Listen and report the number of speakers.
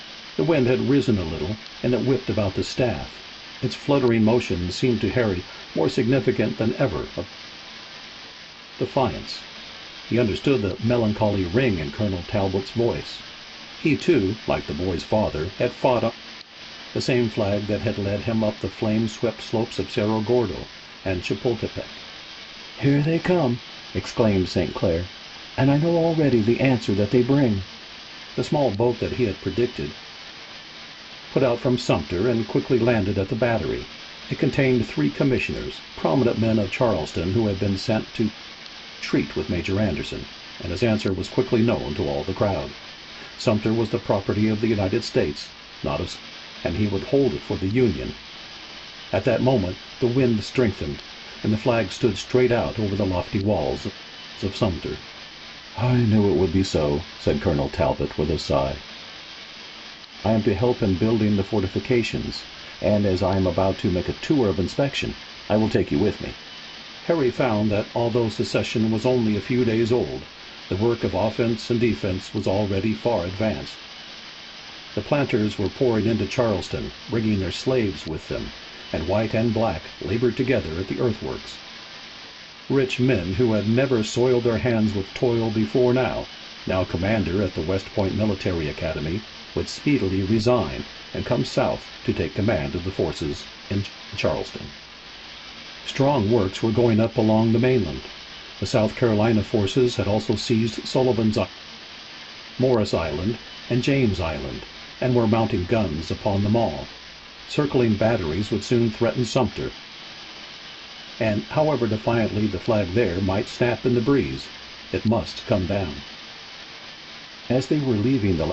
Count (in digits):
1